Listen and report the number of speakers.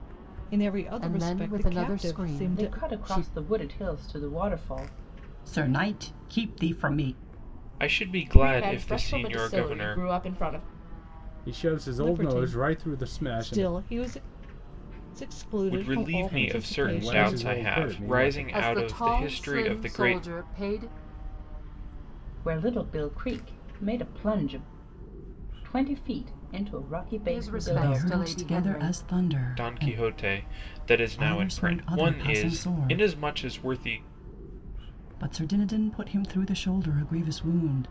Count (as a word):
seven